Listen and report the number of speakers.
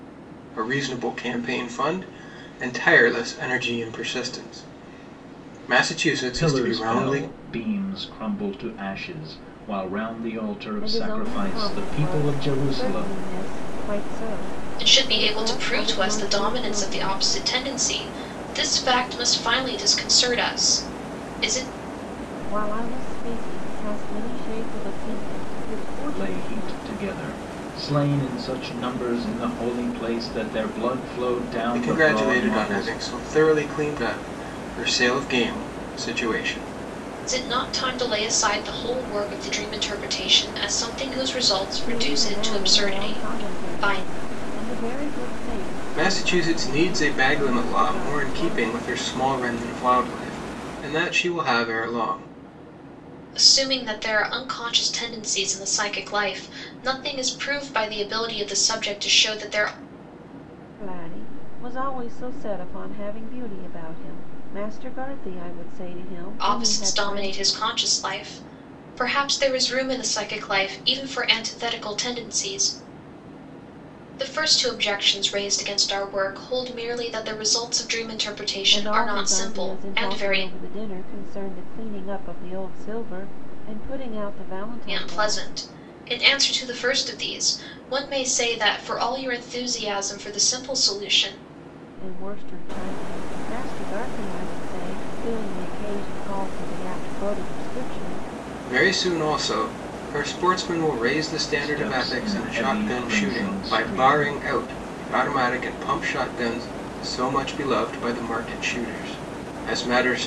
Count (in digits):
4